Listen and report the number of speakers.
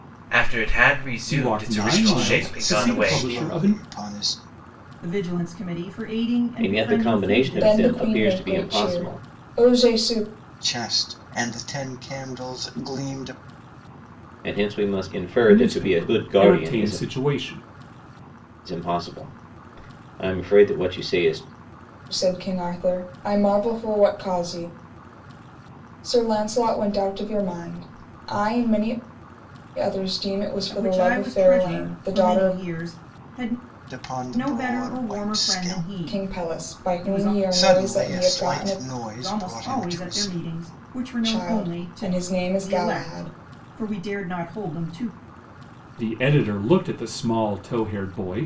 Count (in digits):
6